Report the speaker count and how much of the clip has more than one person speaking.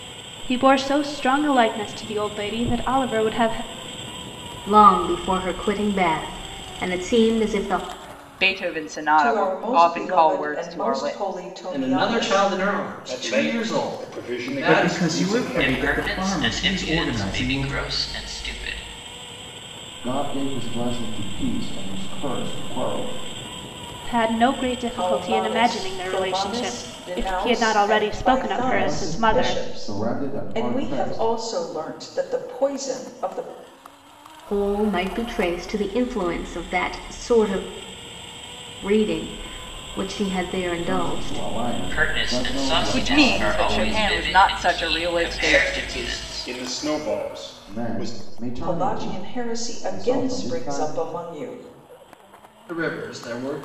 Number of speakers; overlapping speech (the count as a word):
nine, about 41%